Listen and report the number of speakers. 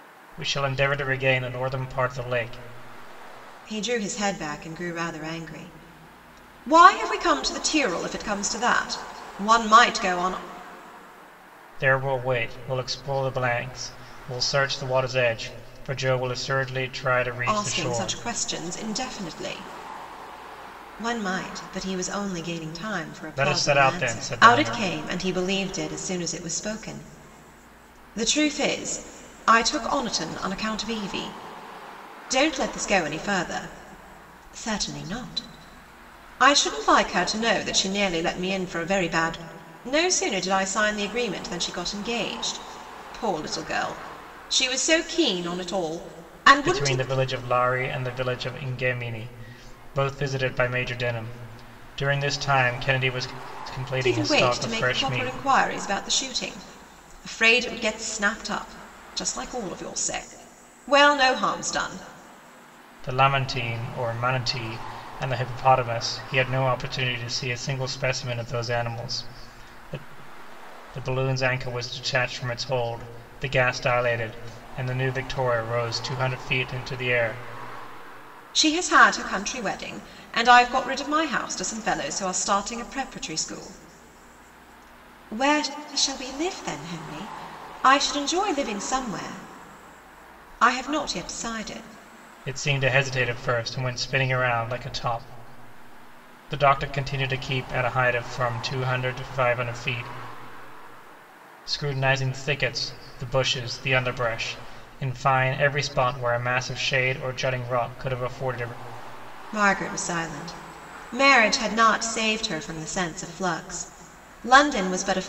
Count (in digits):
2